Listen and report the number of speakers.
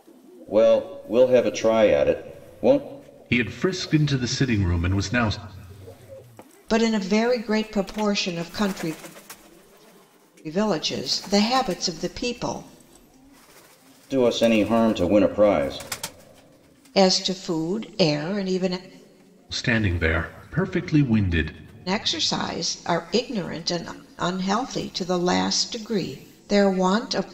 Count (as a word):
three